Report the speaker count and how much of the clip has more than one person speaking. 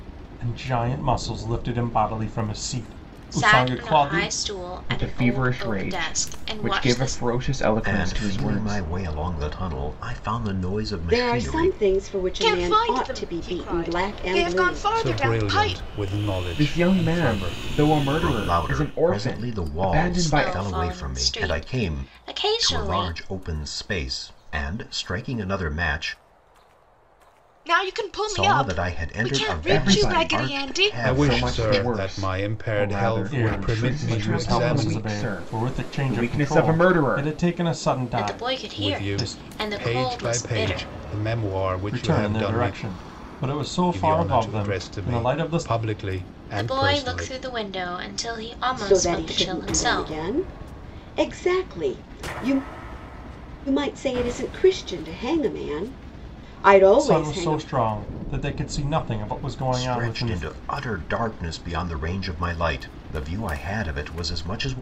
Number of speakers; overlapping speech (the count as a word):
seven, about 50%